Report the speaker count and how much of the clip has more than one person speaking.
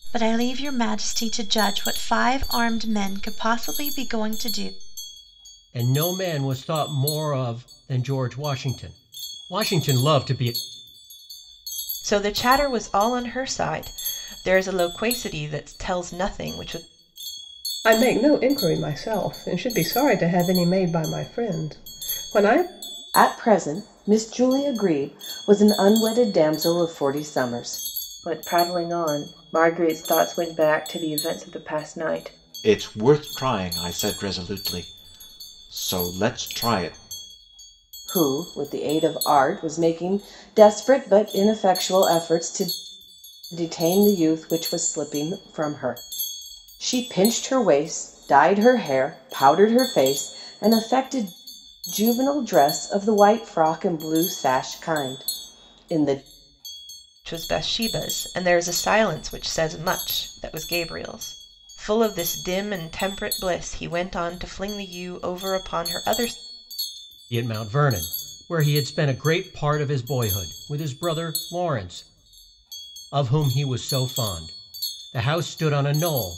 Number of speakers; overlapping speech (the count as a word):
seven, no overlap